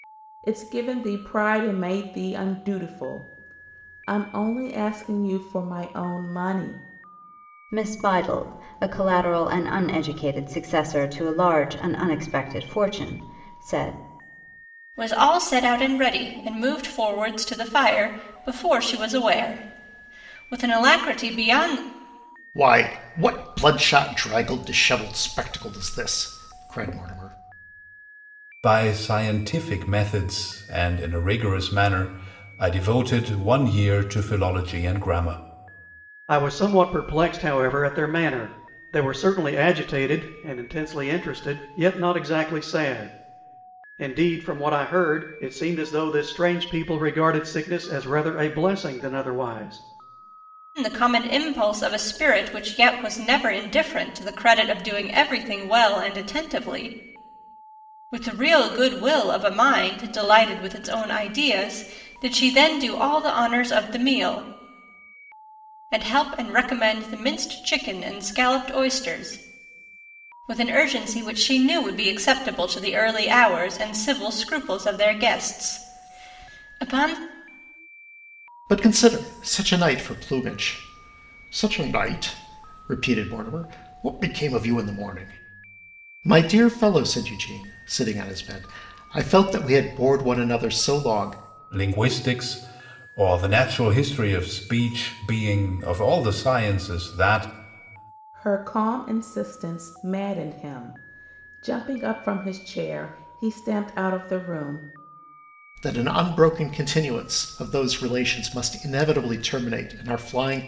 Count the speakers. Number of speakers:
6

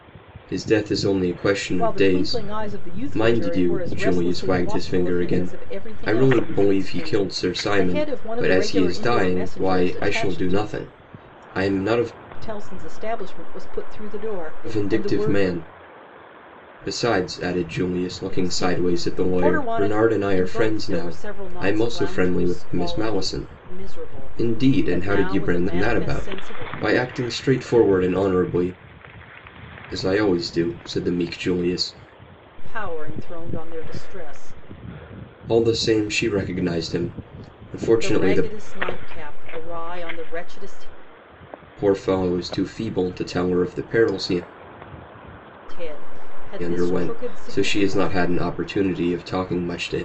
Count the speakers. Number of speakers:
2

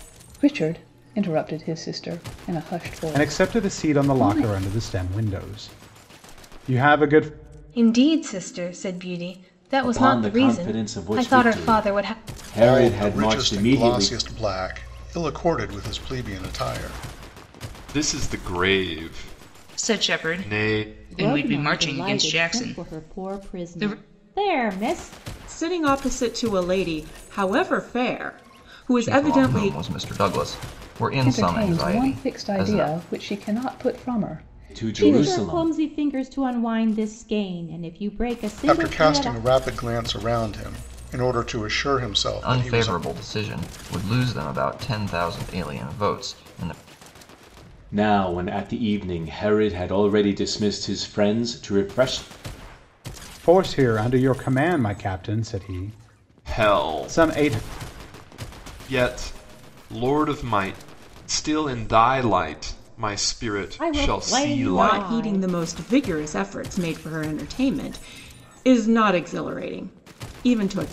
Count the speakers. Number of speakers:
10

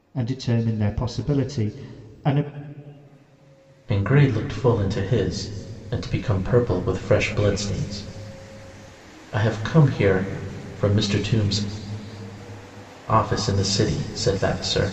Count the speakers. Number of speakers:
2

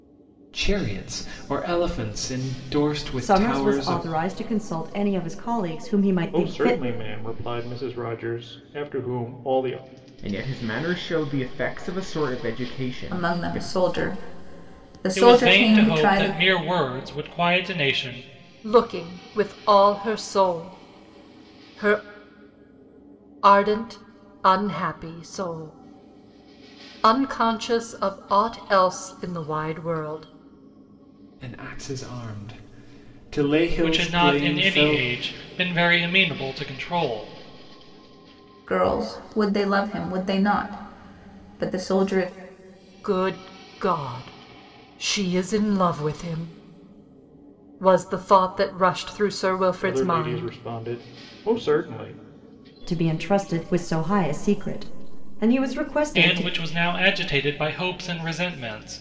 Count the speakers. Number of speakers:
7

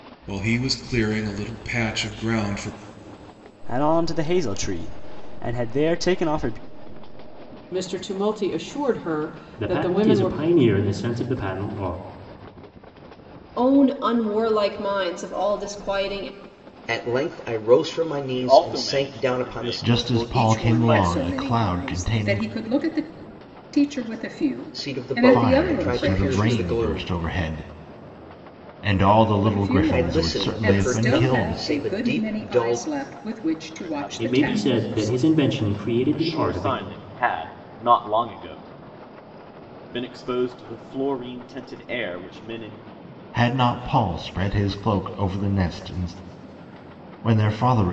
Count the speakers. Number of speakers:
9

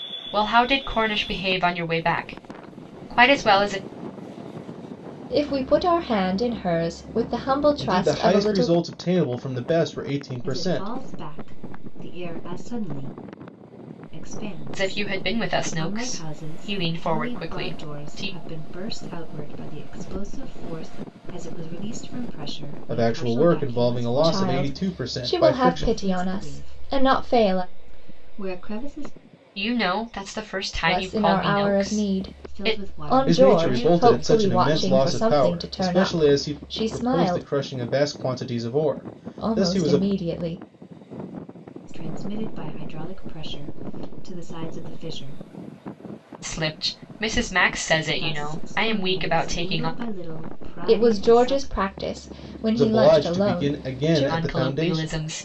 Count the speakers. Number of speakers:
4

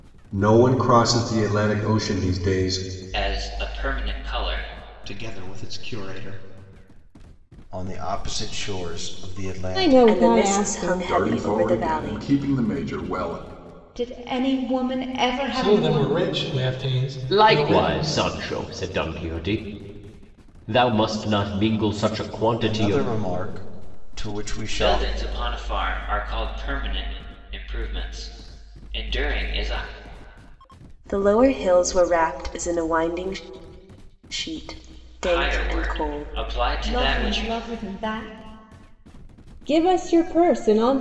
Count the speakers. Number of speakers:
10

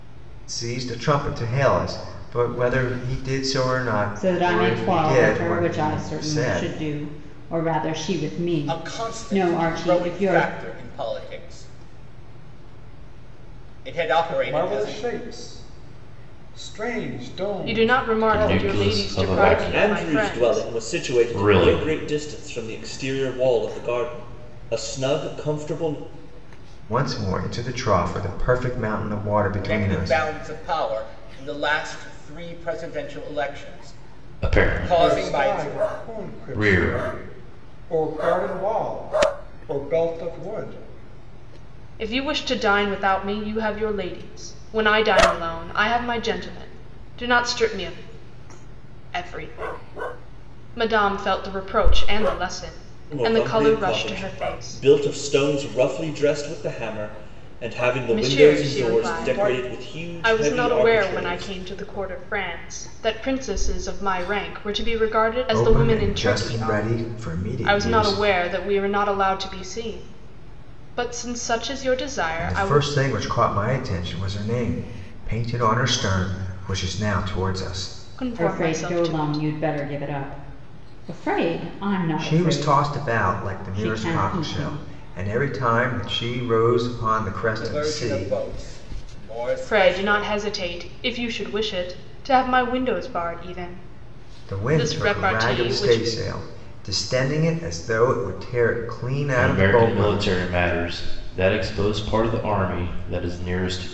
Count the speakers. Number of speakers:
7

